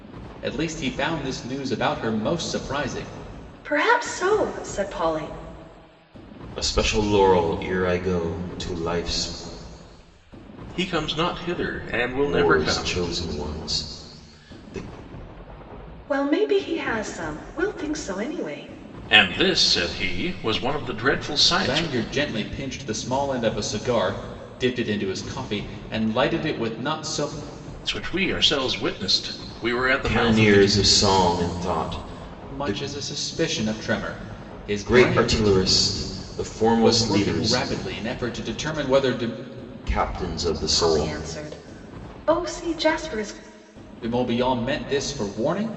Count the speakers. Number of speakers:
4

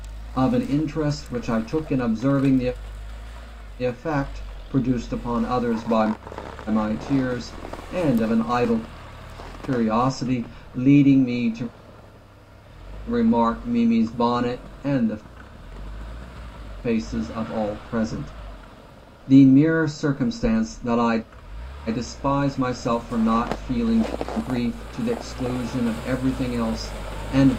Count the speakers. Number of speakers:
1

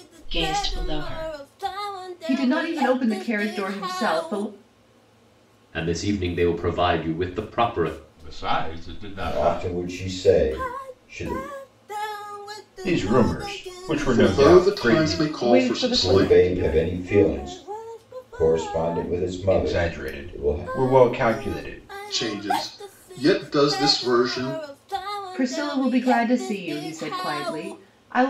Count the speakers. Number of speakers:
7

